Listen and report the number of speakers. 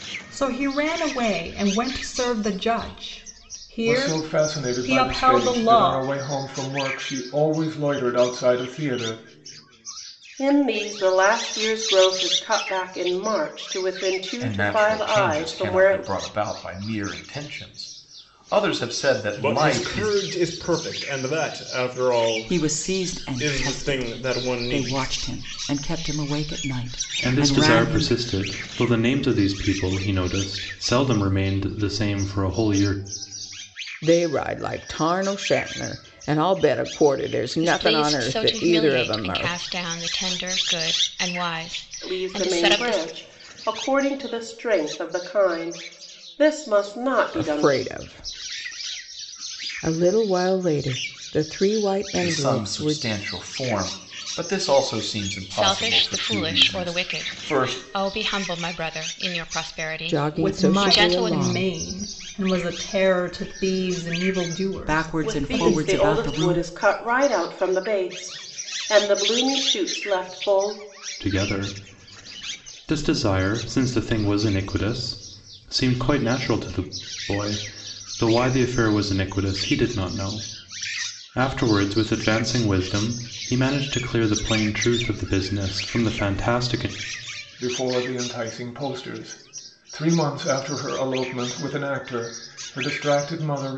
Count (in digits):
9